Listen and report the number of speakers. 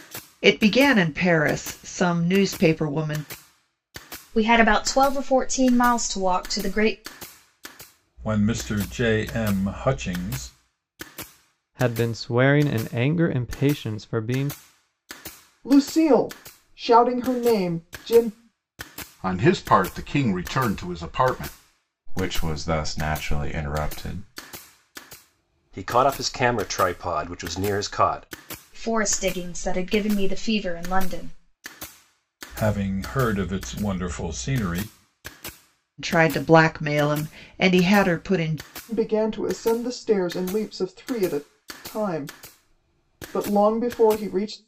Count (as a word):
eight